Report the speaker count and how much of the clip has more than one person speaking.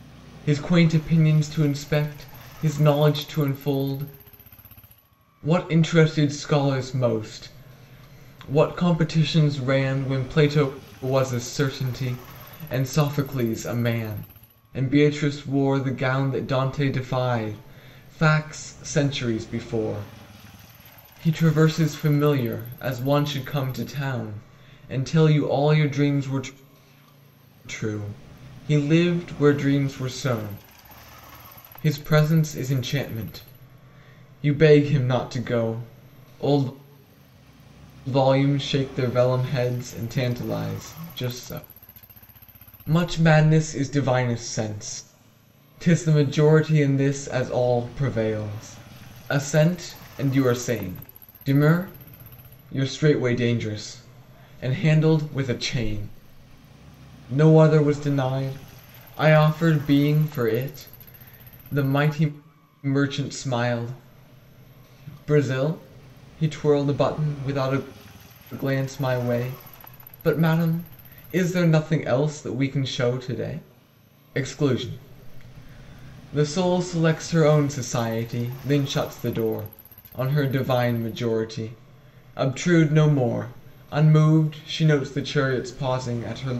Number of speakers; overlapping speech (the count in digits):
1, no overlap